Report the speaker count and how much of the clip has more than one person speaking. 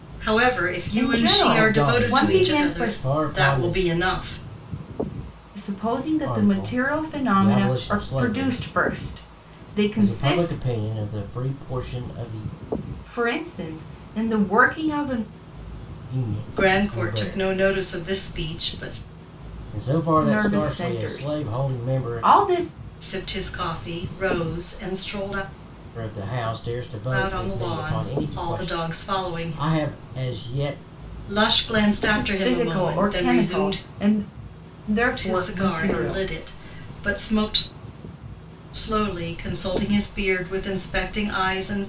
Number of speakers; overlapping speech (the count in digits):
3, about 34%